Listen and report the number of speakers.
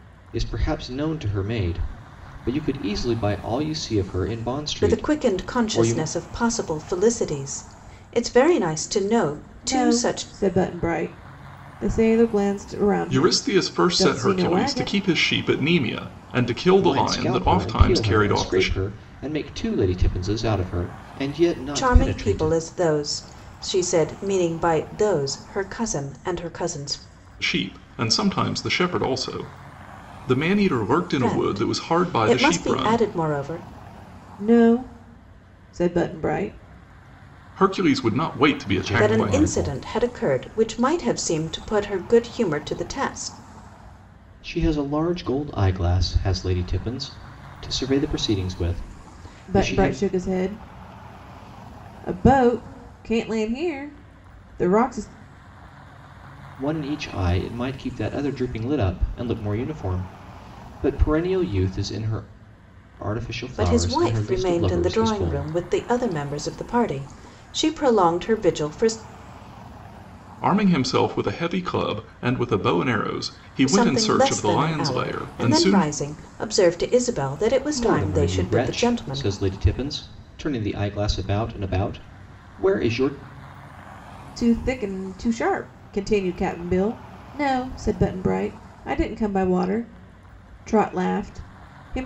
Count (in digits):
4